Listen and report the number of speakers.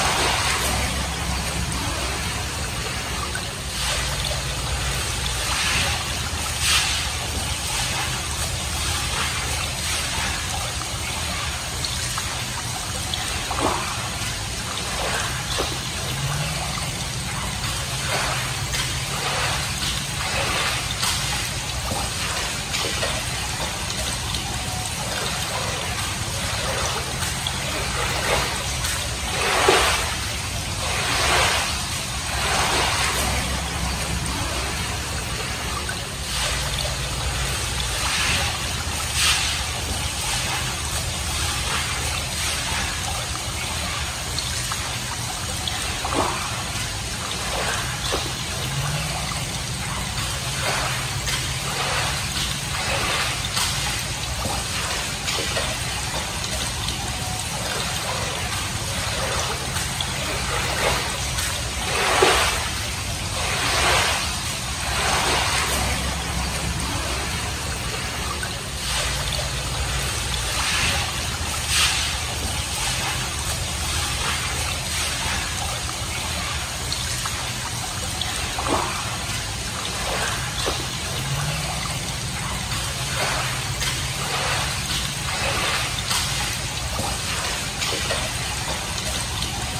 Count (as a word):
zero